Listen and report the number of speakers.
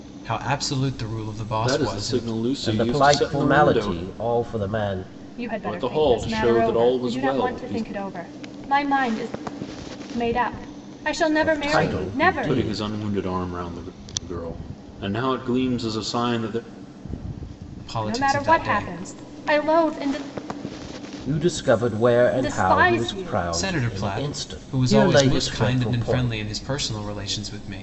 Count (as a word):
four